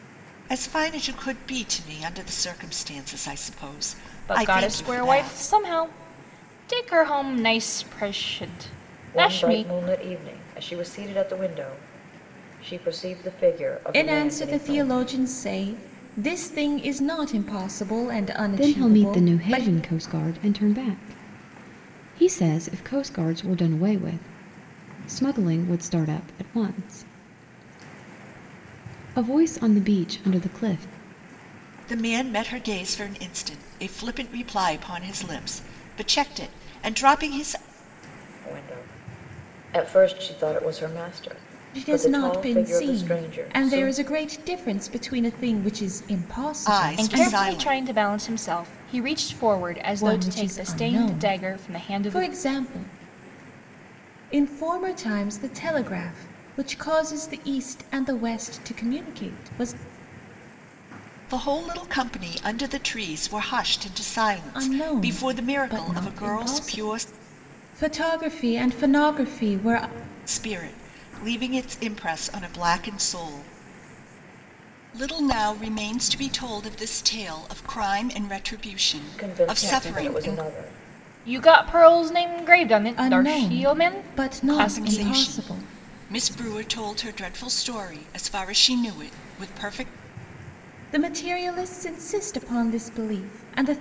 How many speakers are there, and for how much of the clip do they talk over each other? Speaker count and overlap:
5, about 18%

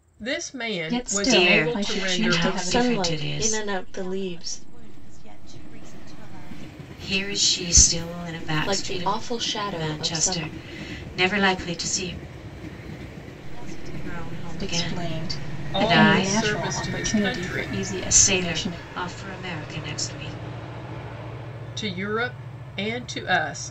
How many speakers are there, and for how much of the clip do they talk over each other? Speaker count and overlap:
5, about 43%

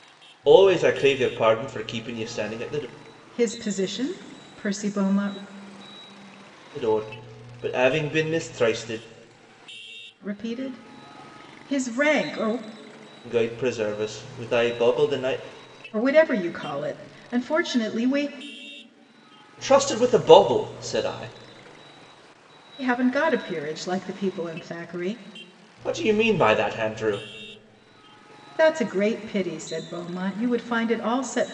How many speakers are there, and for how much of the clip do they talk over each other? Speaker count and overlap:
2, no overlap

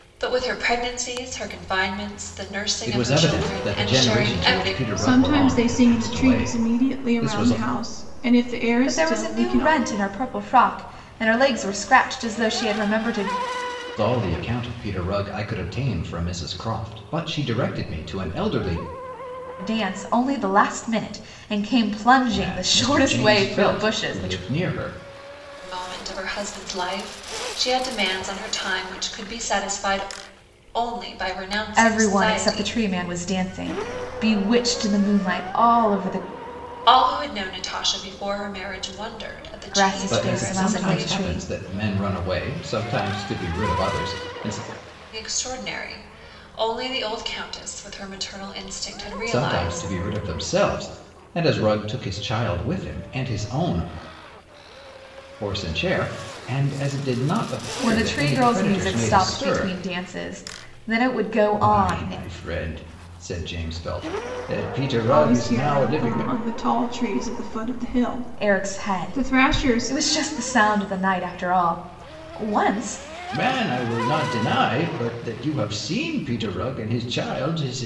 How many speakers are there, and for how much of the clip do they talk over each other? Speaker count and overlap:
4, about 21%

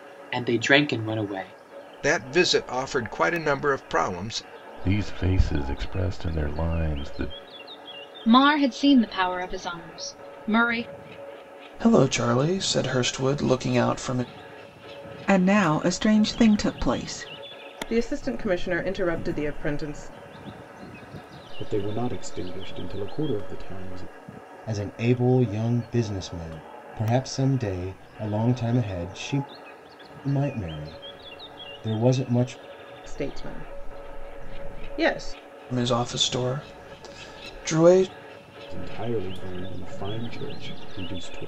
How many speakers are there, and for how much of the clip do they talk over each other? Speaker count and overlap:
9, no overlap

